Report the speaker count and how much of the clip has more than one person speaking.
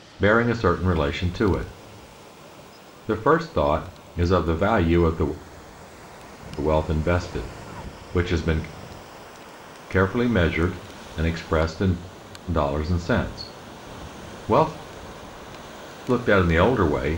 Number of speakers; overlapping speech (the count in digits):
1, no overlap